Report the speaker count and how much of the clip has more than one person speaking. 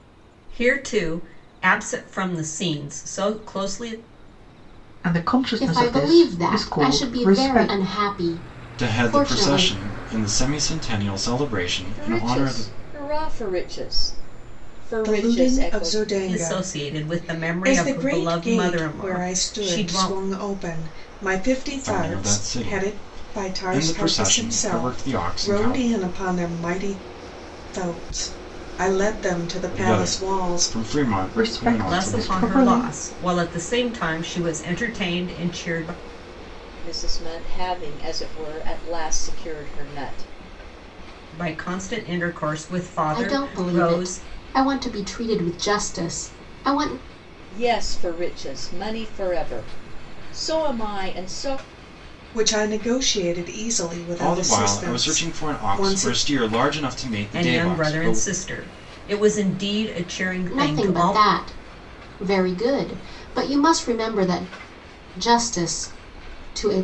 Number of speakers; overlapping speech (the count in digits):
6, about 30%